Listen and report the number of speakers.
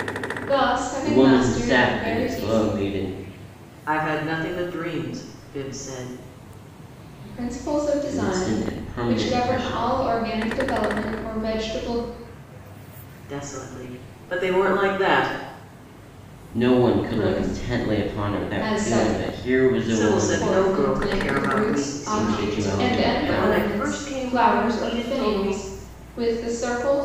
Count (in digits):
3